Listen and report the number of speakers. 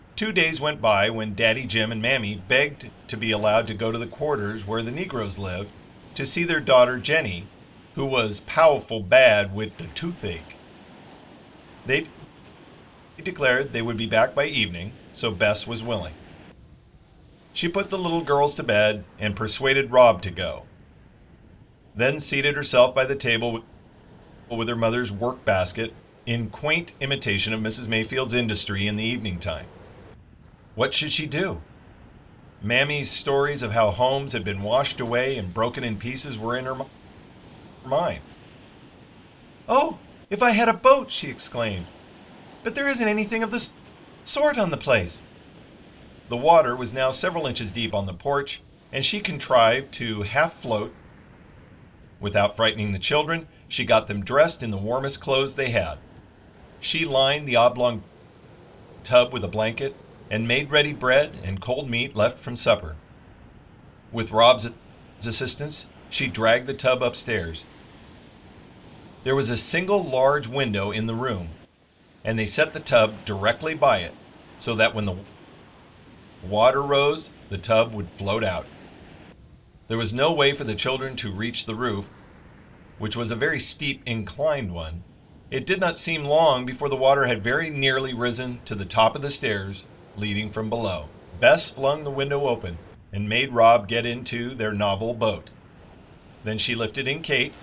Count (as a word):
one